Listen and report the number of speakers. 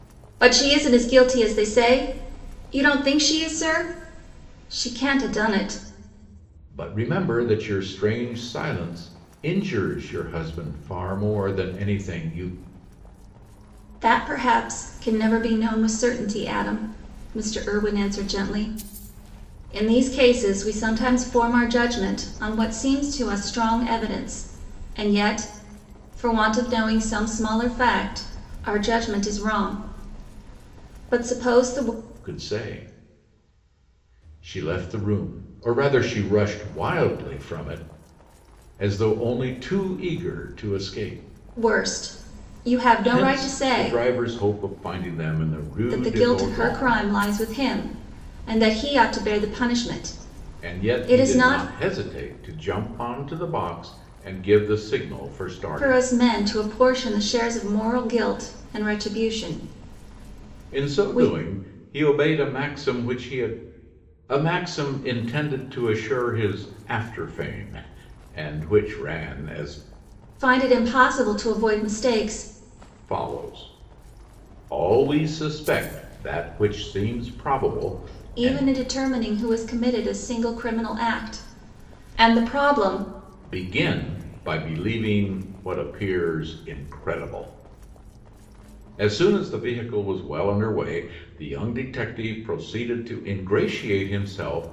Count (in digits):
2